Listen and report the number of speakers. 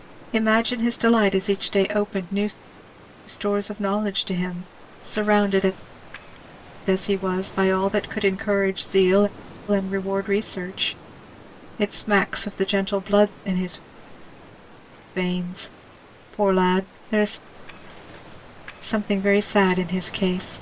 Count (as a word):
one